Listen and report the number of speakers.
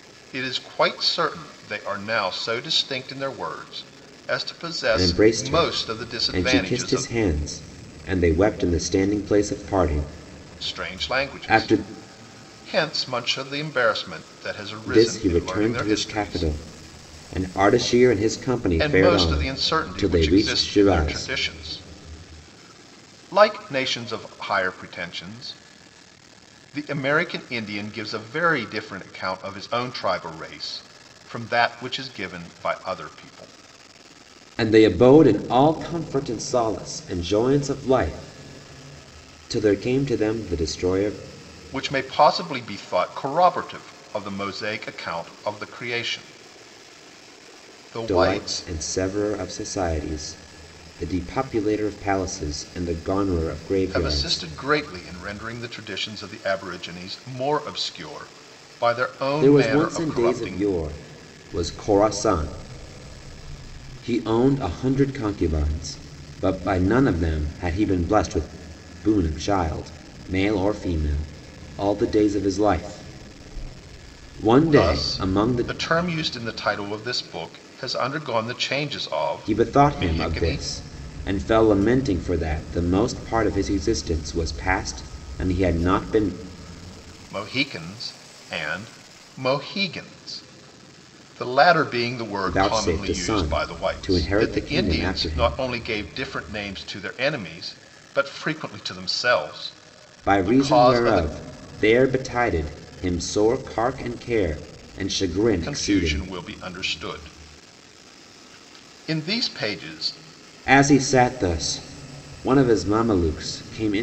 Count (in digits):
2